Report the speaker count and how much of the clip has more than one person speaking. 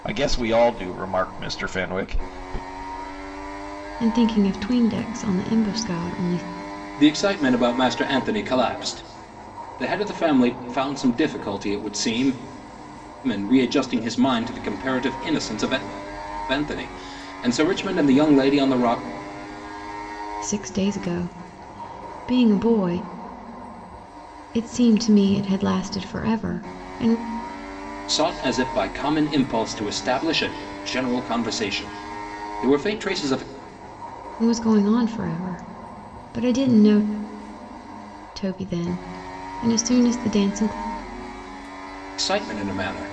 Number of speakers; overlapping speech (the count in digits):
3, no overlap